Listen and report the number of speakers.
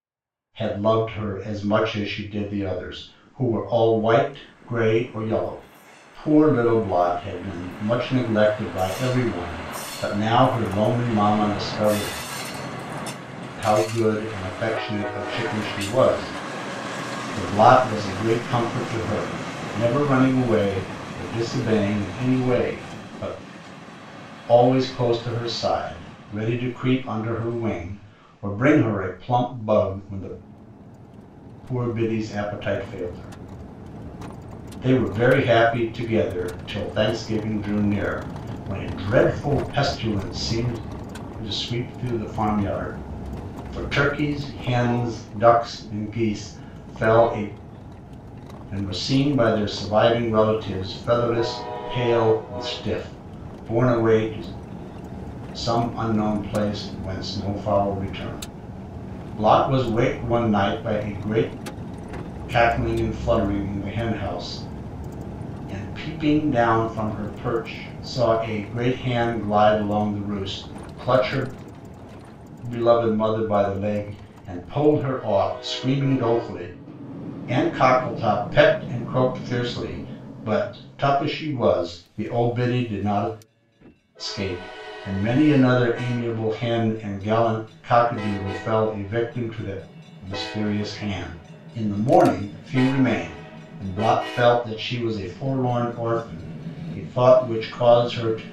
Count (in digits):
1